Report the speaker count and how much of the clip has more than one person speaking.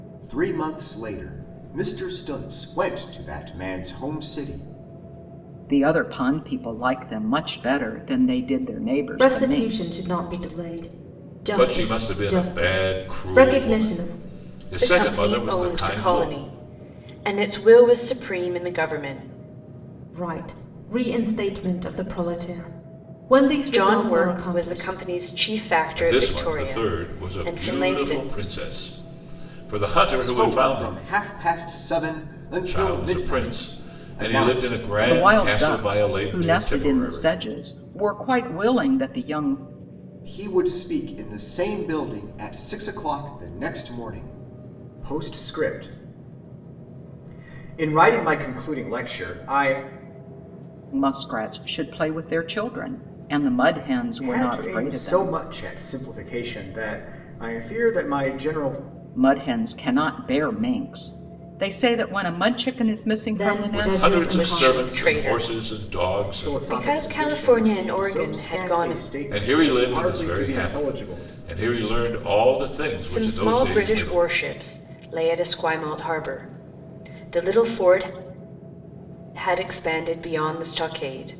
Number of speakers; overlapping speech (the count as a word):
five, about 30%